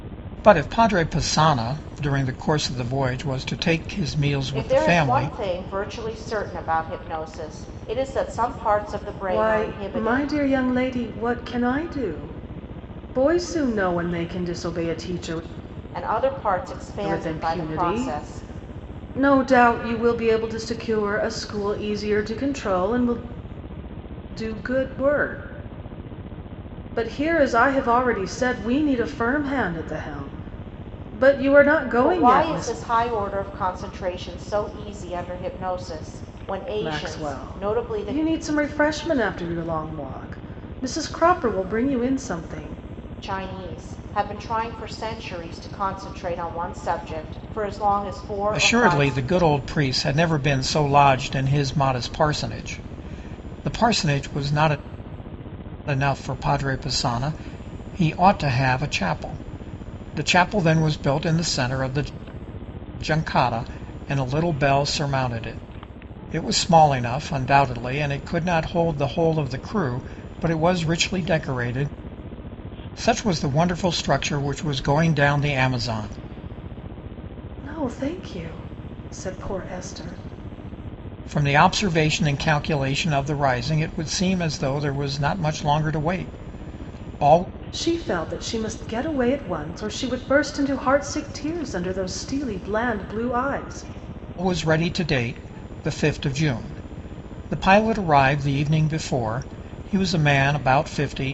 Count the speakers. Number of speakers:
3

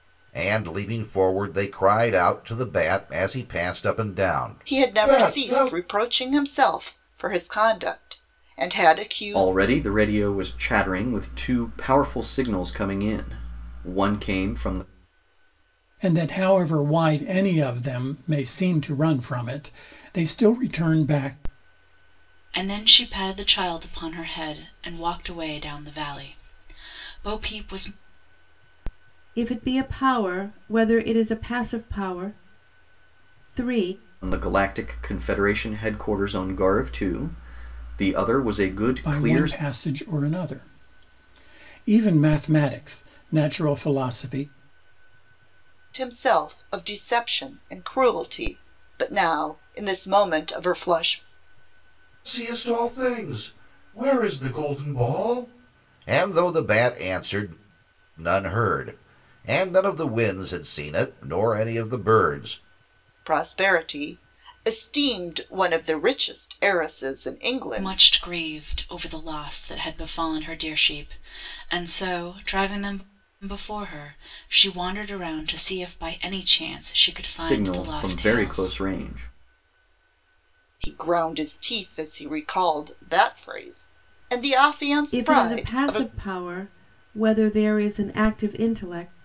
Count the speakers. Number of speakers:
6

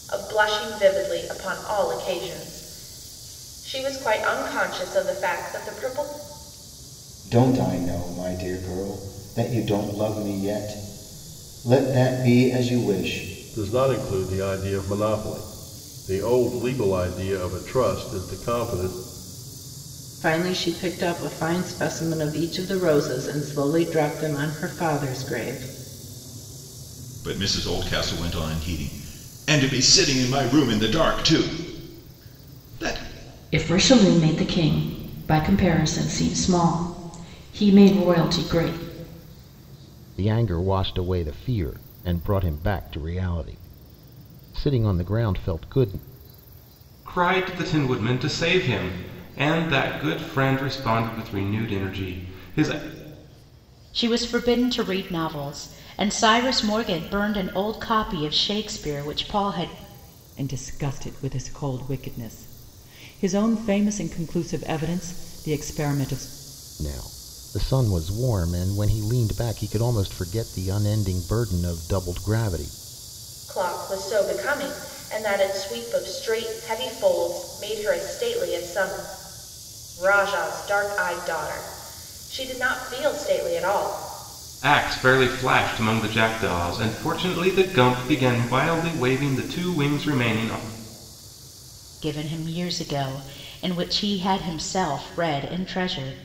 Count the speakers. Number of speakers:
10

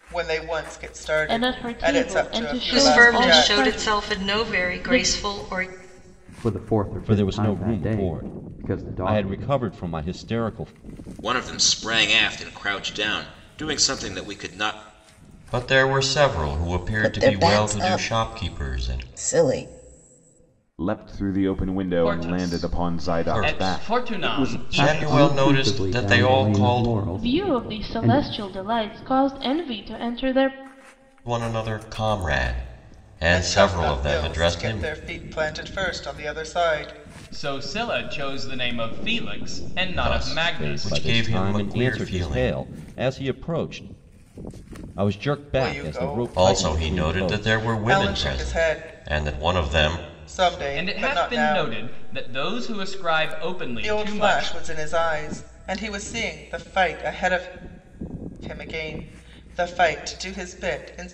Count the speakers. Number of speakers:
10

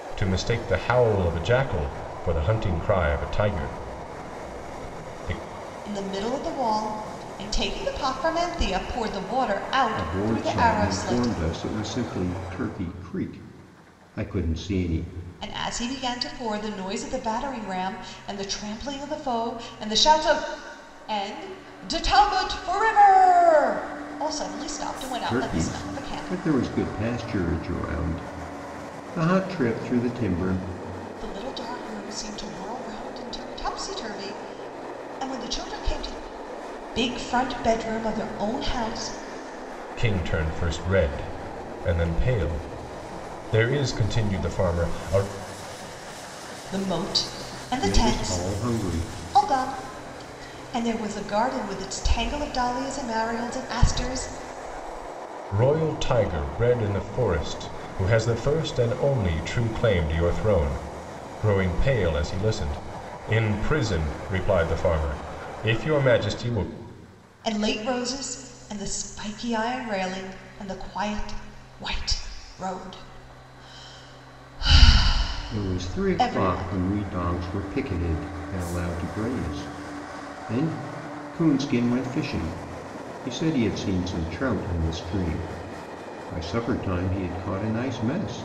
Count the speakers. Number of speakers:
3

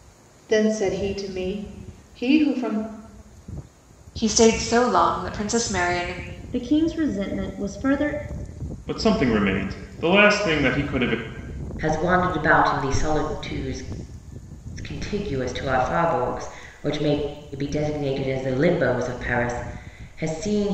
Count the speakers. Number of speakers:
5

